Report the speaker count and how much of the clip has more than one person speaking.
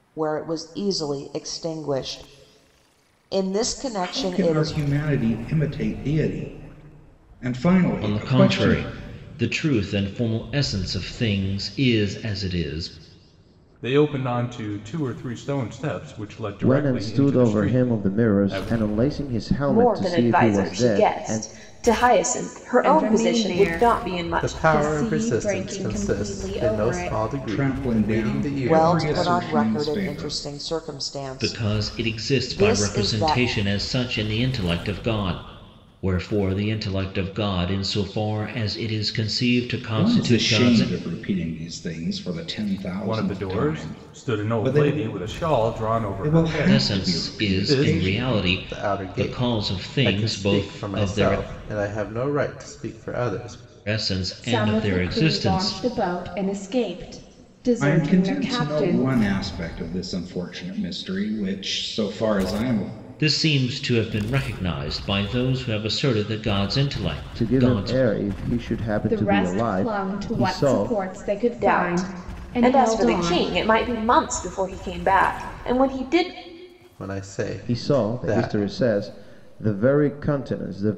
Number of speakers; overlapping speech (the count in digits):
8, about 39%